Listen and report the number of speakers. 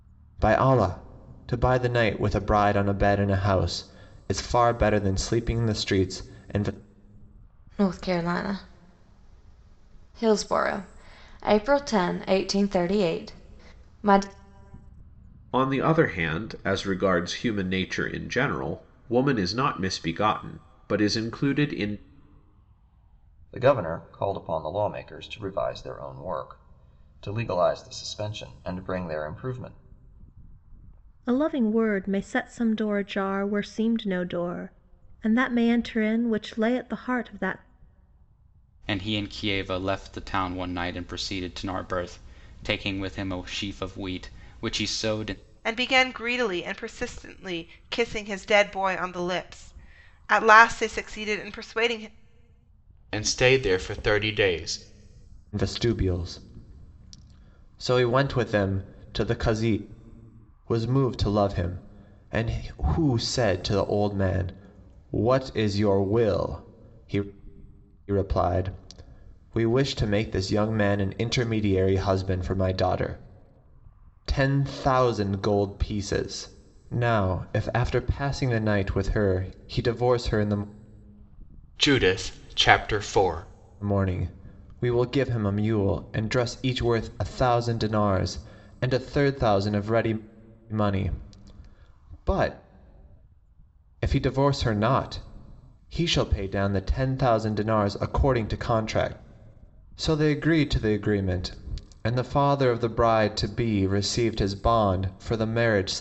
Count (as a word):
eight